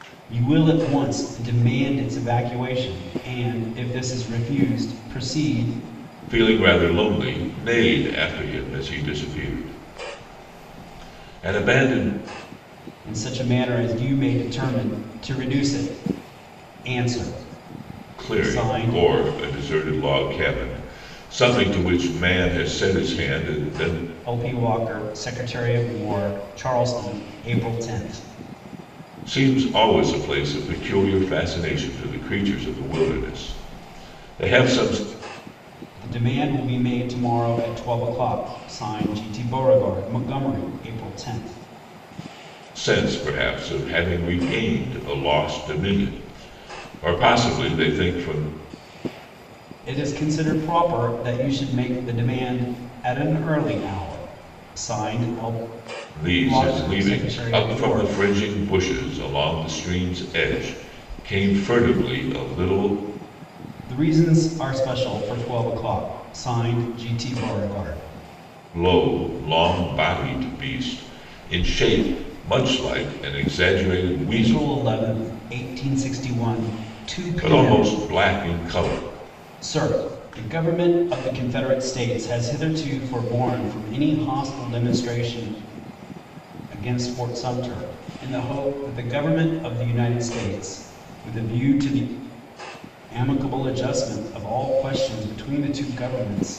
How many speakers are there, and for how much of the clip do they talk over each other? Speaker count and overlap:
2, about 4%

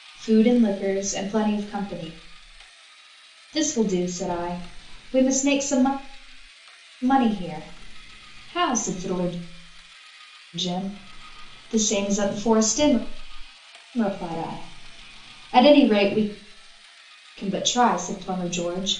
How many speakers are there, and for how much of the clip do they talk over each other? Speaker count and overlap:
1, no overlap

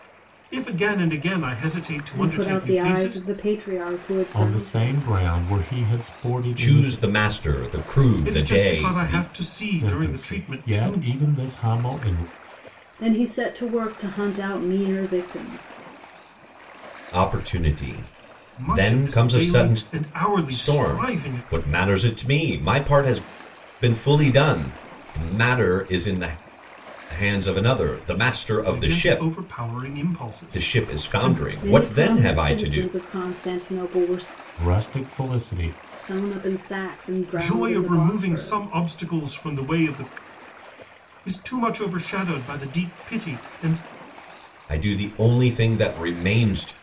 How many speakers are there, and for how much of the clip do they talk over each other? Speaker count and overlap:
4, about 24%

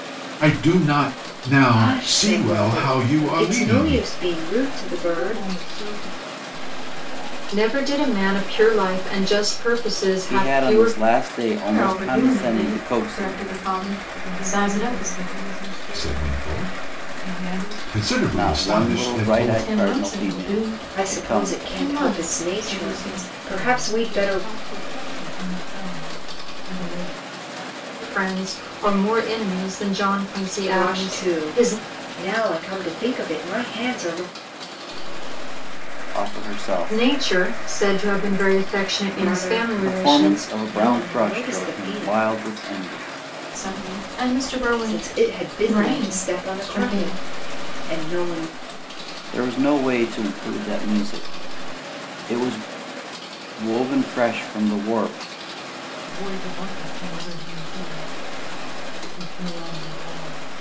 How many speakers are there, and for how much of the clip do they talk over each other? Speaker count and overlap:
8, about 54%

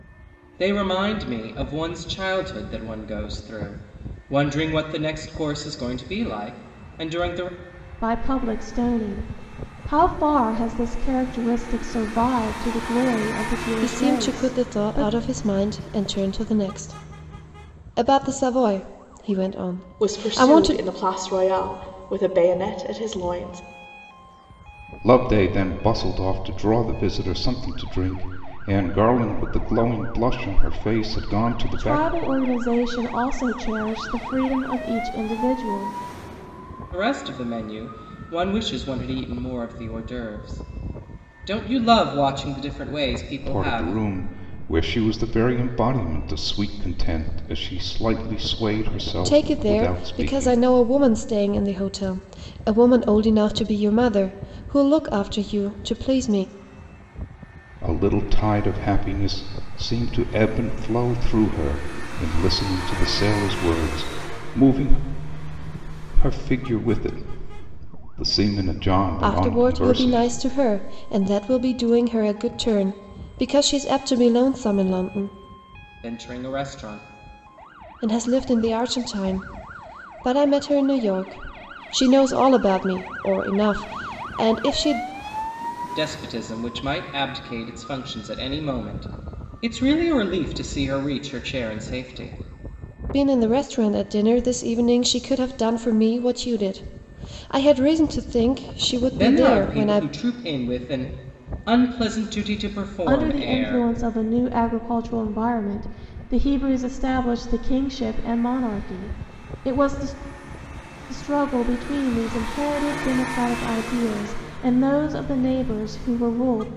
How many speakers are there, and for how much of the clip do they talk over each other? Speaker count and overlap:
5, about 7%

